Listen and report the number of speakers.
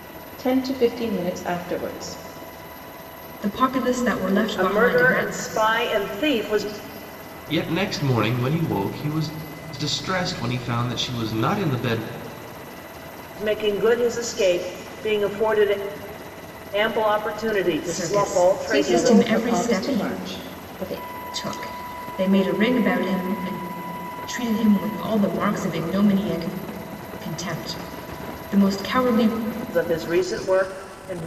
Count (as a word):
four